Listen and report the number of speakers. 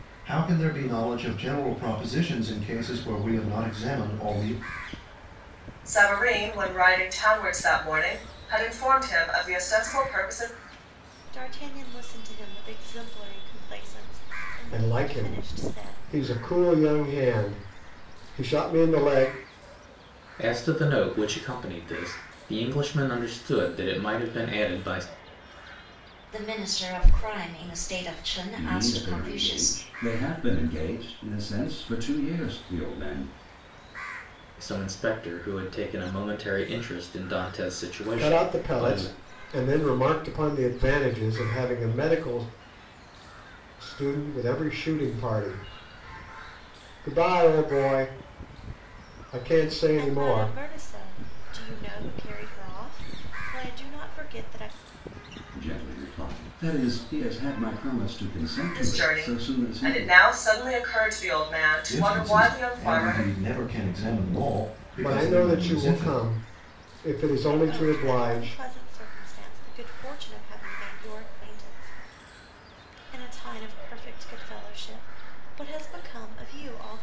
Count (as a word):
seven